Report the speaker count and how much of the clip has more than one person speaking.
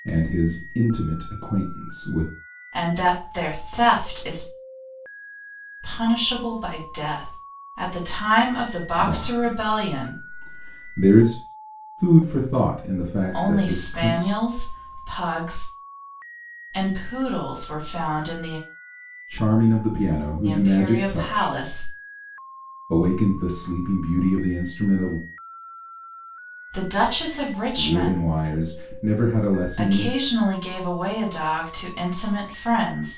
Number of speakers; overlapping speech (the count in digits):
2, about 13%